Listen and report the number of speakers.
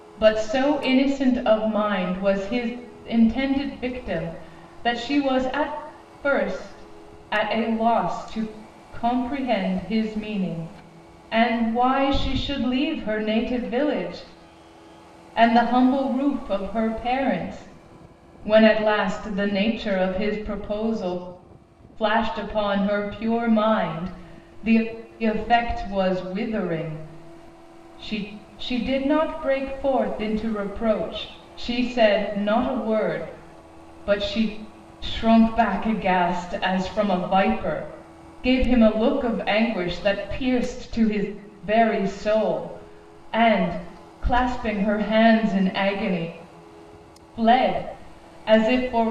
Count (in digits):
1